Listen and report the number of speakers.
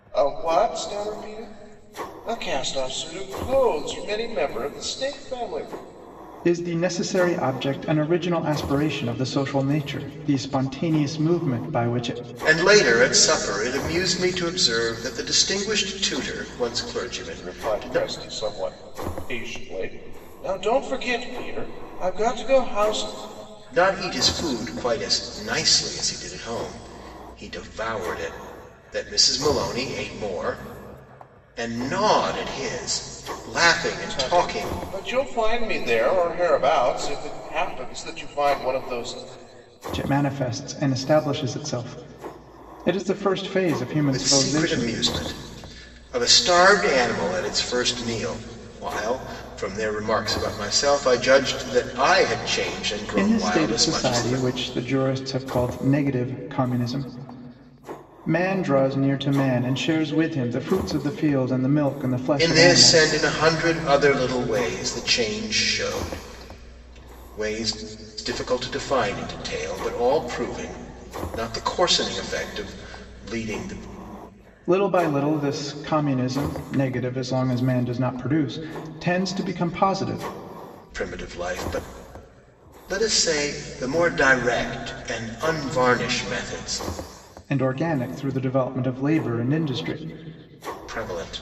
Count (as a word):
three